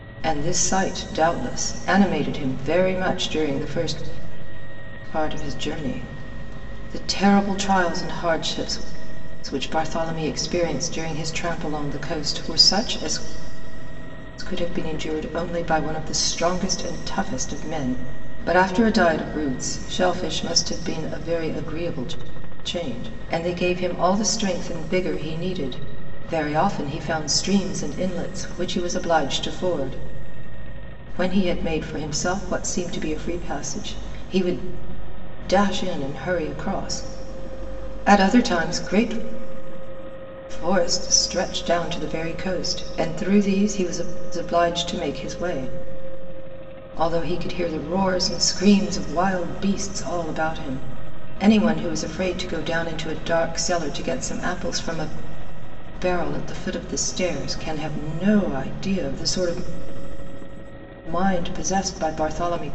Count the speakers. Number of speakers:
one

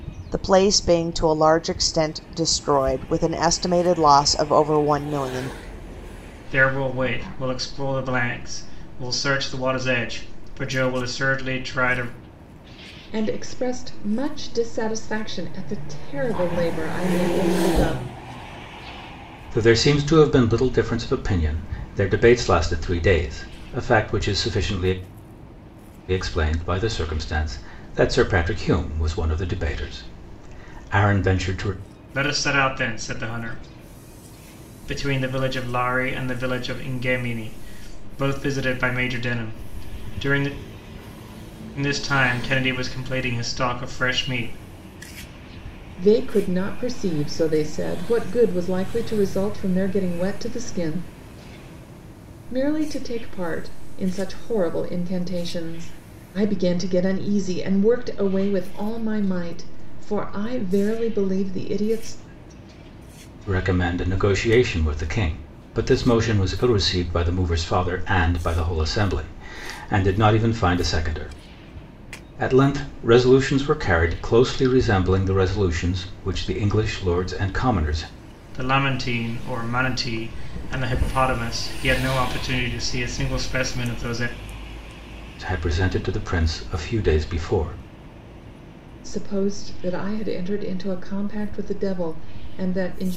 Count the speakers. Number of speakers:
four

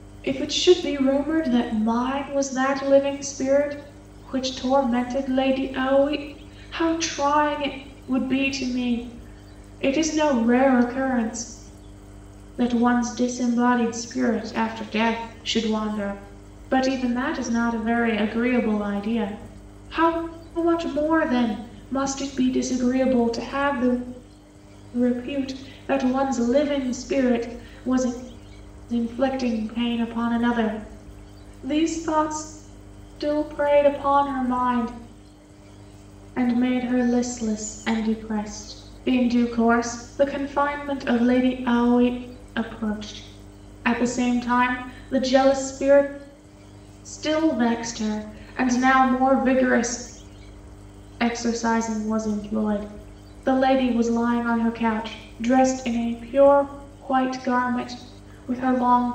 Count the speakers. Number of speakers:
one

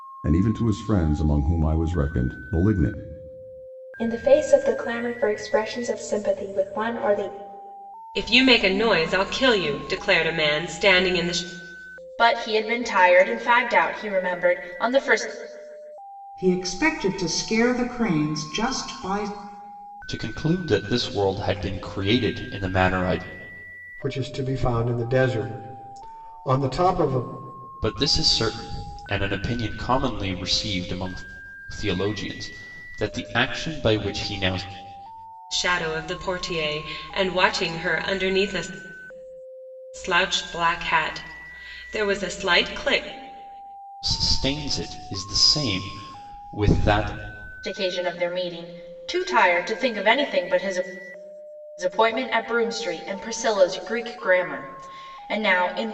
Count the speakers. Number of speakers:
seven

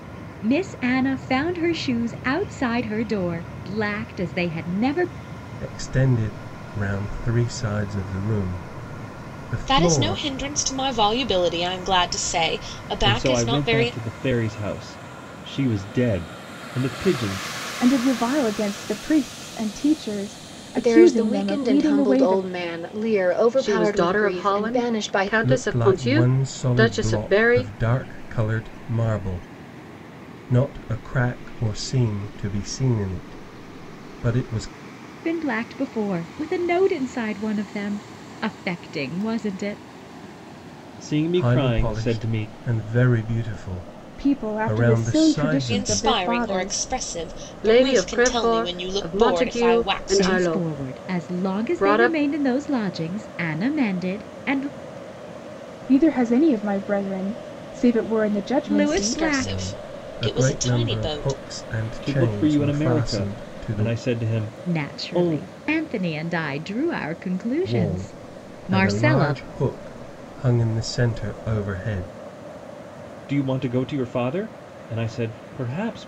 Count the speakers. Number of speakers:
seven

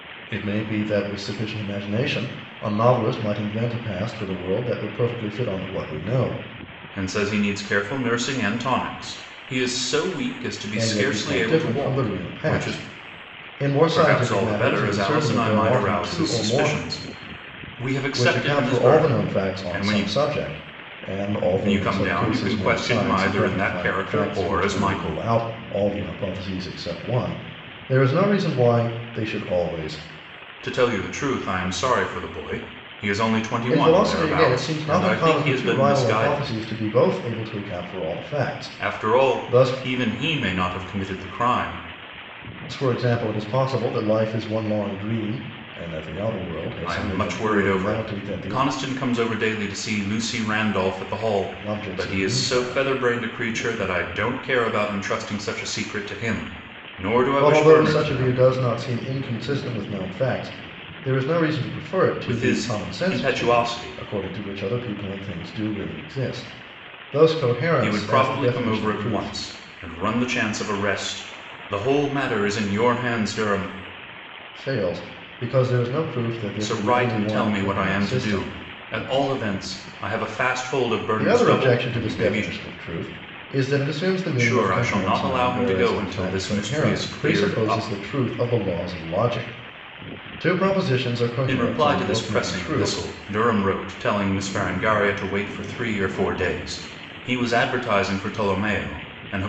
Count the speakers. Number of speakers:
two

